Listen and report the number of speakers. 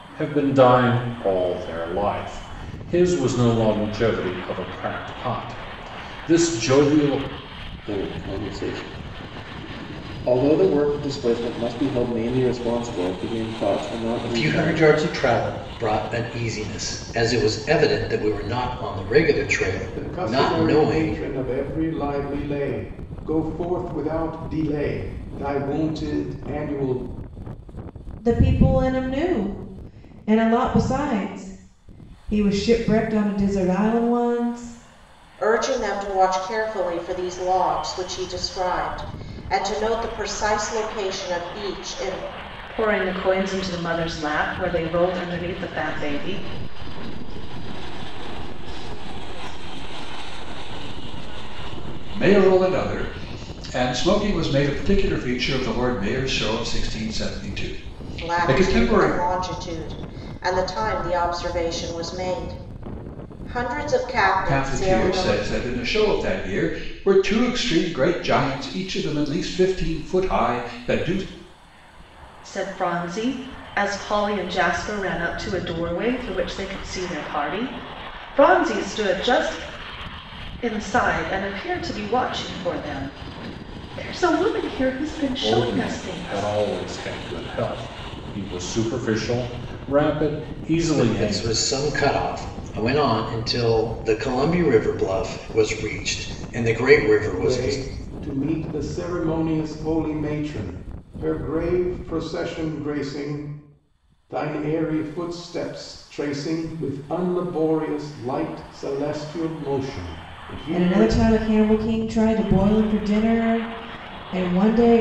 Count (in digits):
9